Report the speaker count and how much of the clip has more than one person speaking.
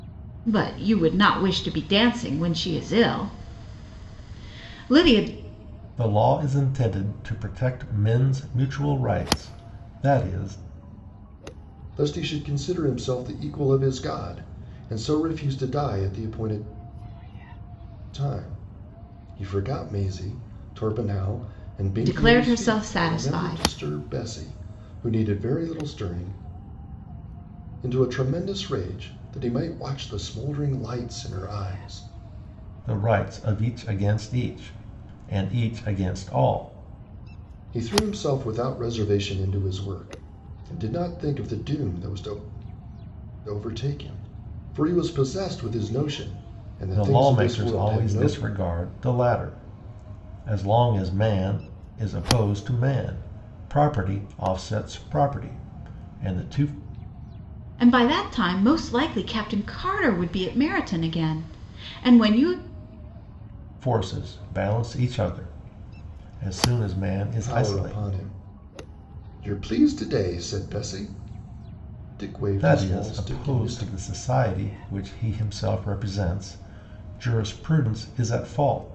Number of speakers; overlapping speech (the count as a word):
three, about 7%